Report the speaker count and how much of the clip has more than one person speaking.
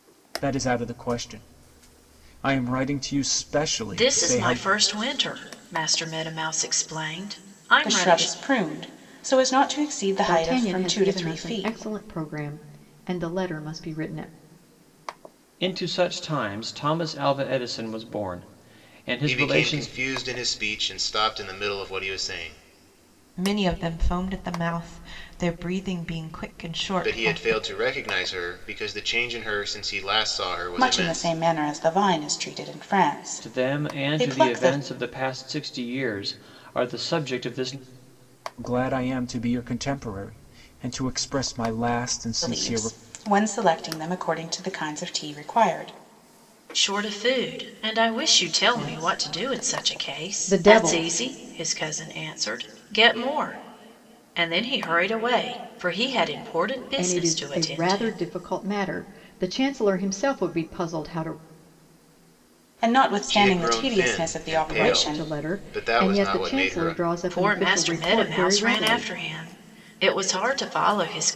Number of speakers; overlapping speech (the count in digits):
7, about 23%